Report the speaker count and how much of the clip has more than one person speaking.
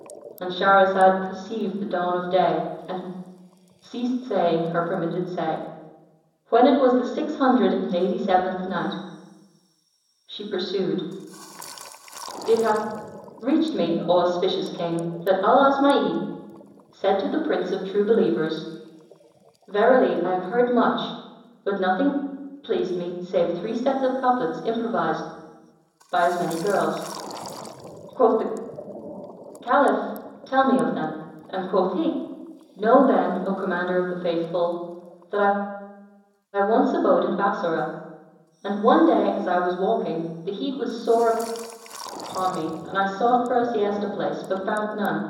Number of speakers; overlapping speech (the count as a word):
one, no overlap